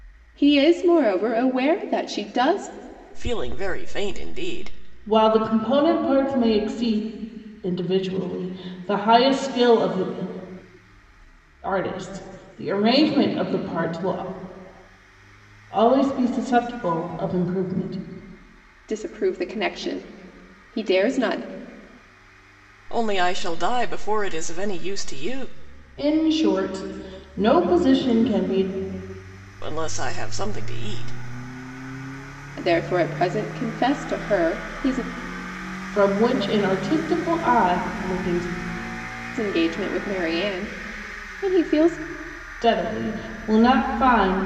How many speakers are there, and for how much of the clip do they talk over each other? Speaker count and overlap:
3, no overlap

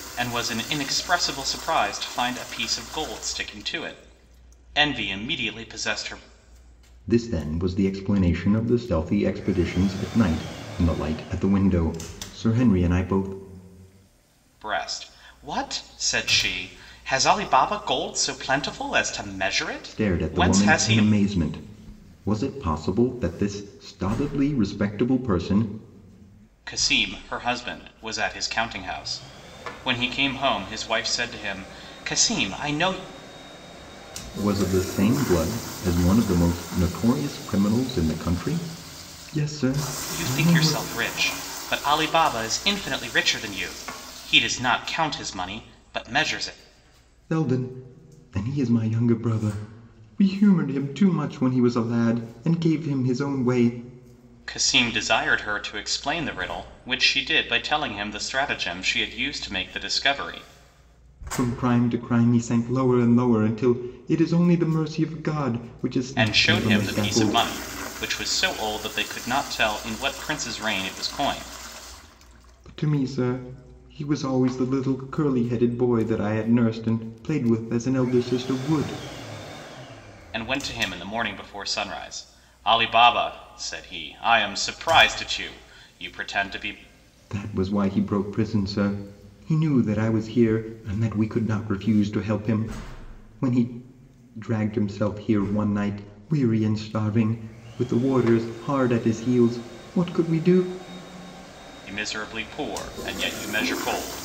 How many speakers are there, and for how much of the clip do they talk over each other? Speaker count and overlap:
2, about 3%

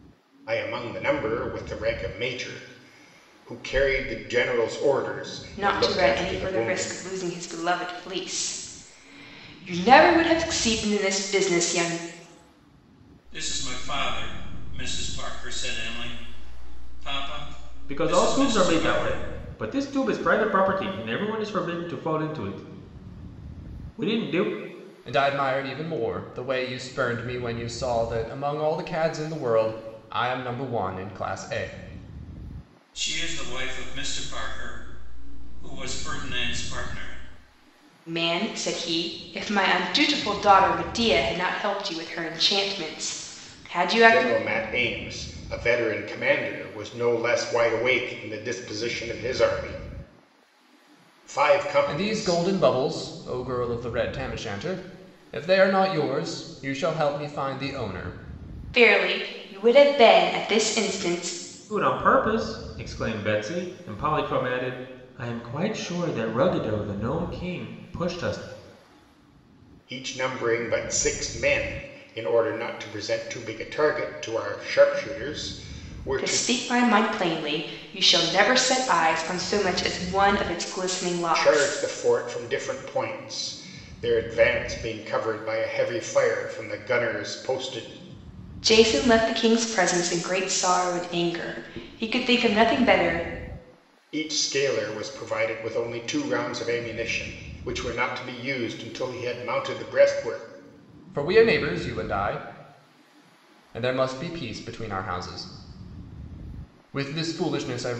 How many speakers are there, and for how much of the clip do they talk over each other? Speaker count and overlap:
5, about 4%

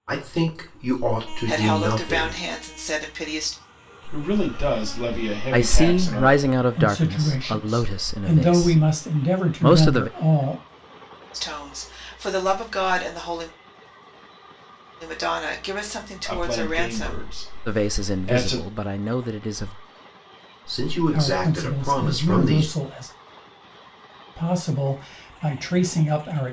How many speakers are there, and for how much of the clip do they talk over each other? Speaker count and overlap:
5, about 32%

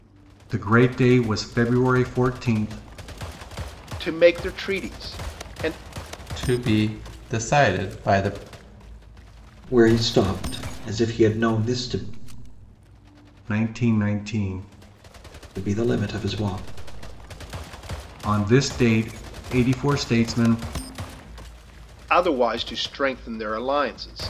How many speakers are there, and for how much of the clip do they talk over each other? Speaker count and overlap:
4, no overlap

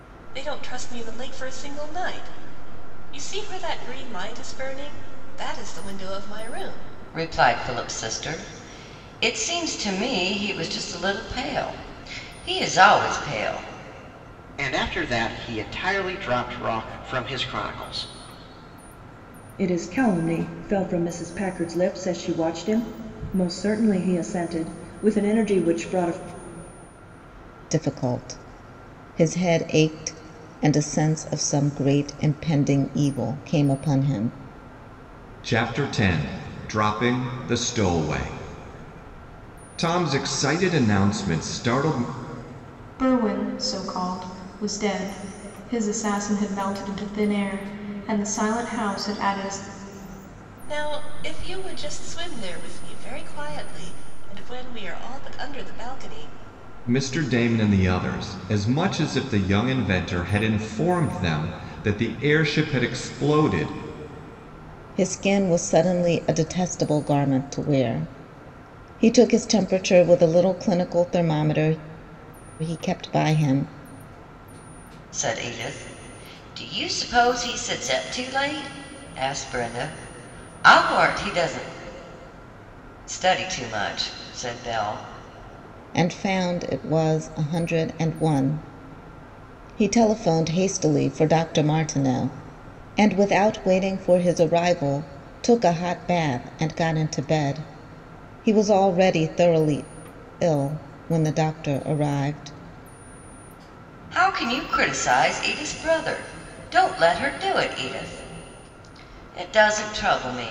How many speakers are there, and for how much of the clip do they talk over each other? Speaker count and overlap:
7, no overlap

